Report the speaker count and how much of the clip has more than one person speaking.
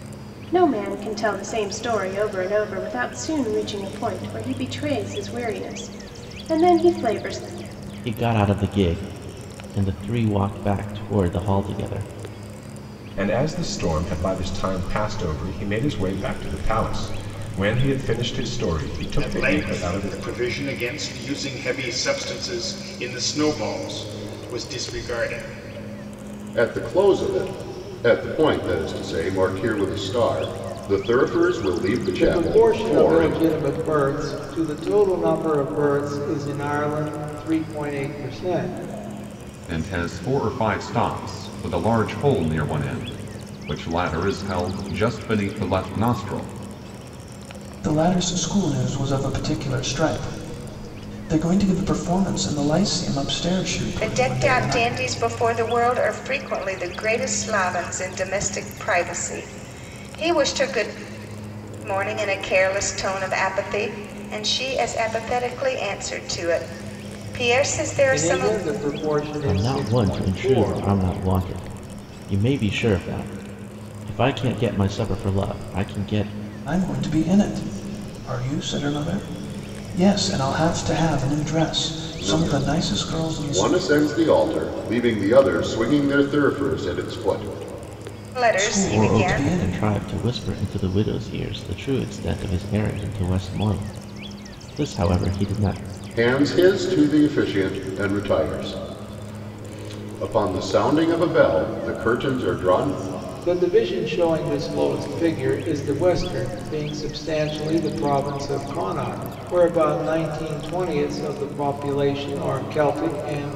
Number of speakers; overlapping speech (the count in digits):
9, about 7%